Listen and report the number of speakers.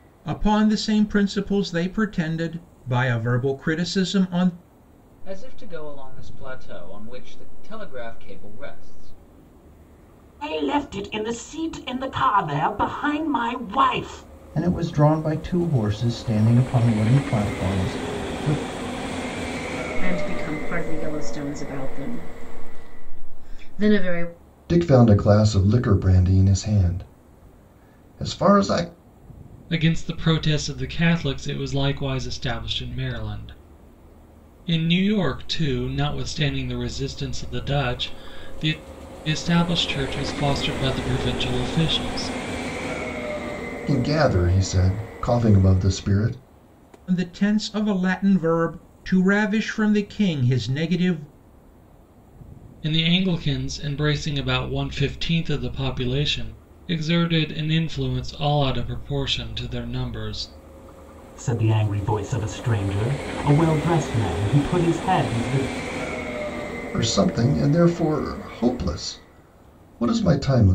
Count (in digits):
7